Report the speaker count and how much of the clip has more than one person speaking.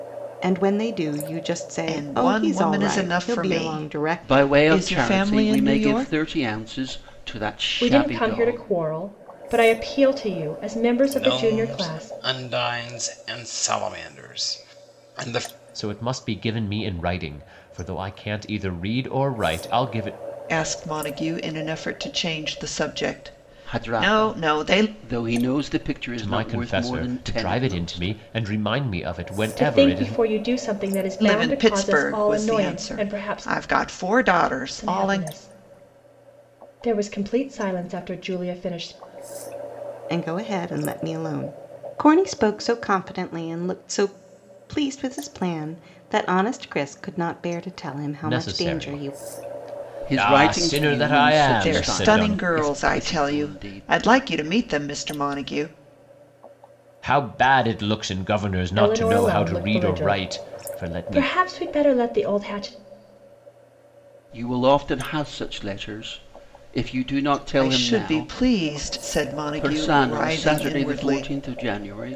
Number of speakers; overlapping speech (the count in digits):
6, about 32%